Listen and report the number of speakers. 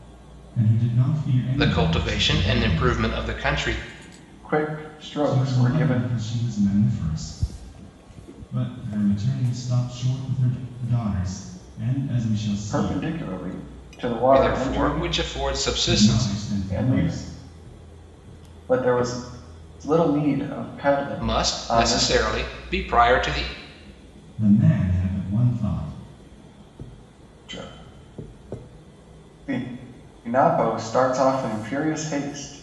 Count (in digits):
3